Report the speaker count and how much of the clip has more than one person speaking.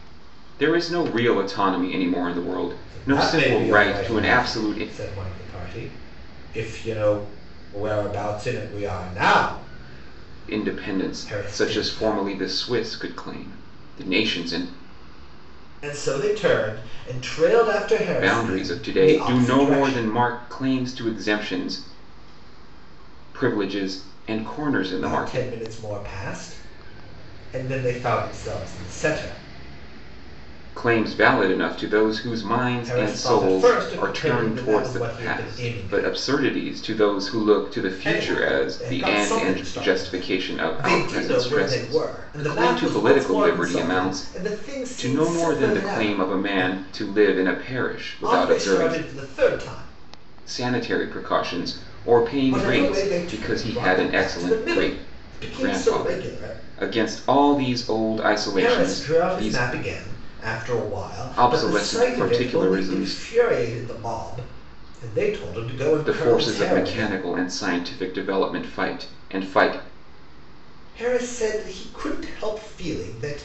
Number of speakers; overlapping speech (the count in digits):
2, about 37%